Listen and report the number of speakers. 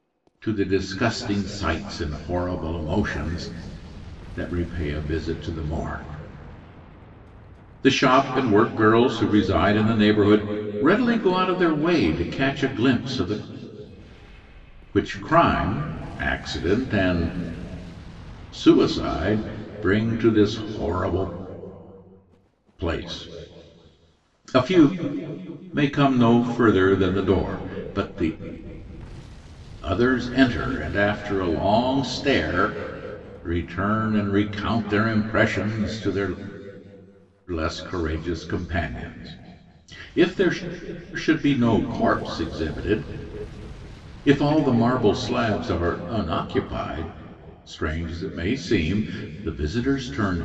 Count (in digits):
1